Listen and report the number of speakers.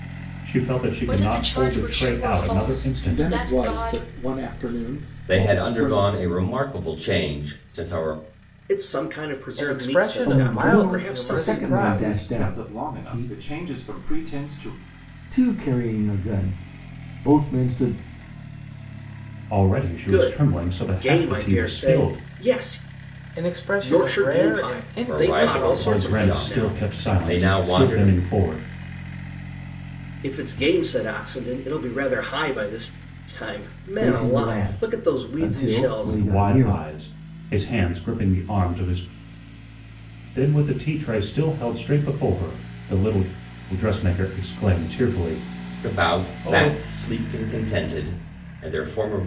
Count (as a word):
eight